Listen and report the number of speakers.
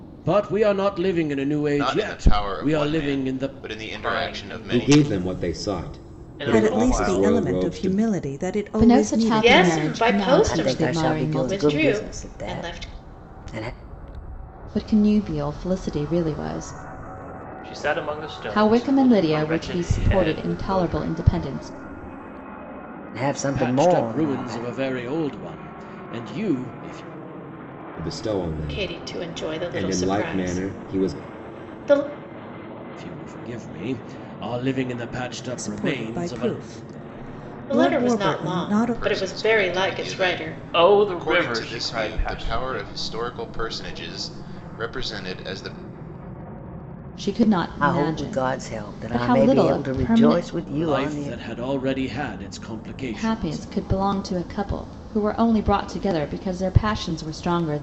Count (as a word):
eight